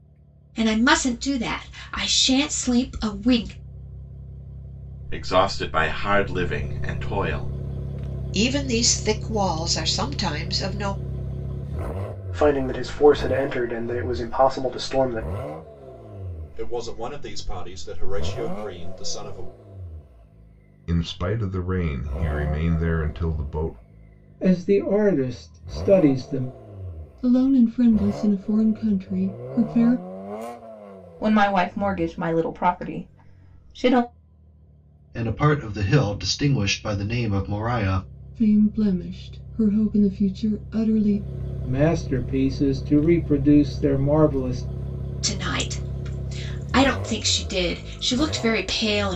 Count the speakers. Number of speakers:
ten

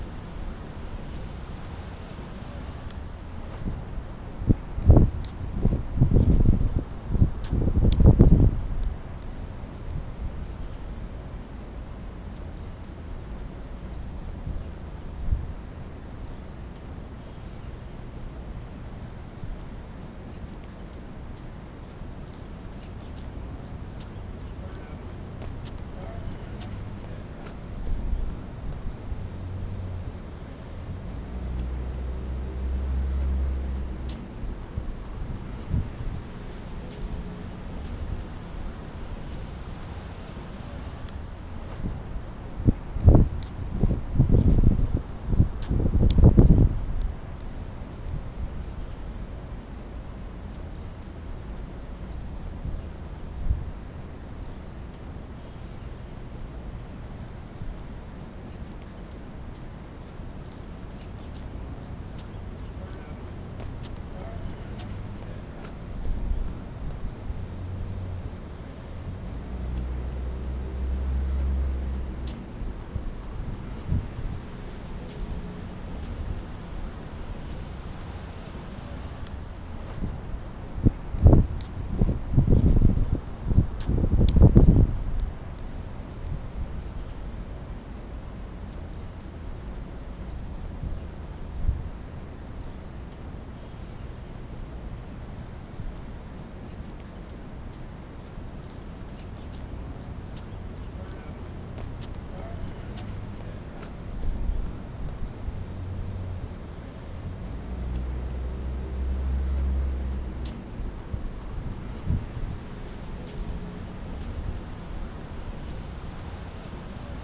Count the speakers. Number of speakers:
zero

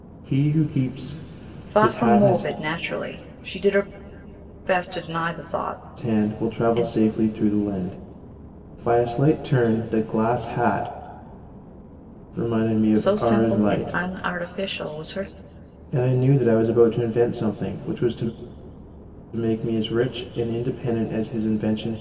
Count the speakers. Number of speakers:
two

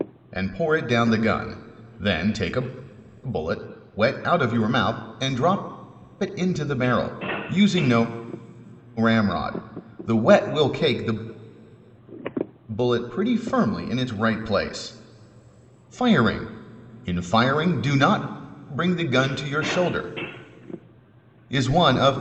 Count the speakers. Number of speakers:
one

